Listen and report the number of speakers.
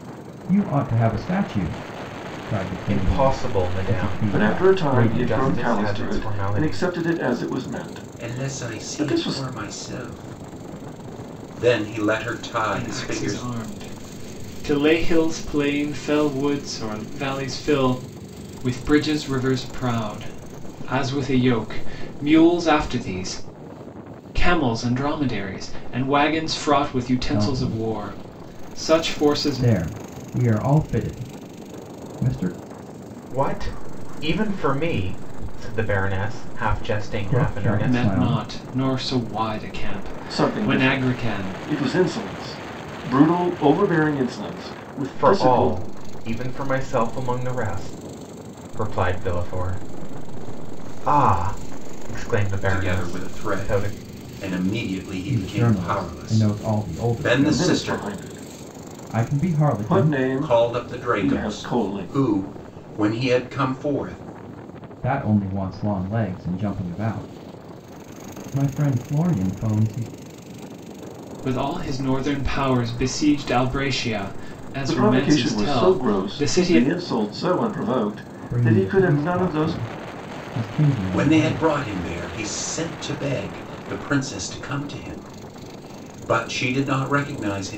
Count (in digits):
5